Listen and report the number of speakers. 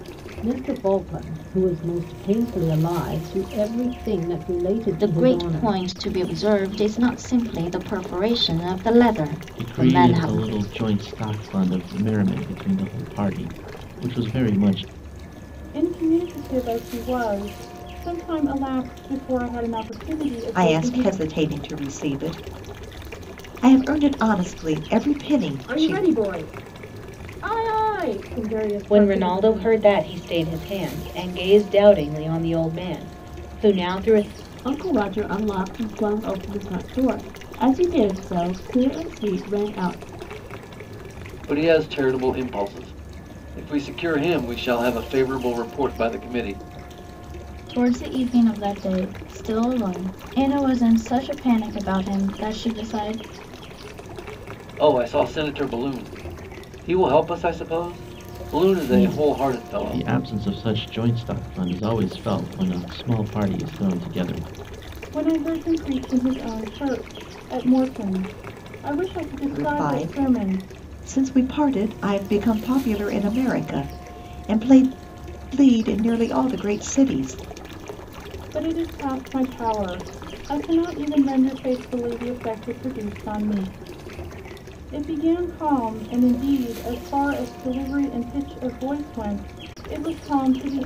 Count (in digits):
10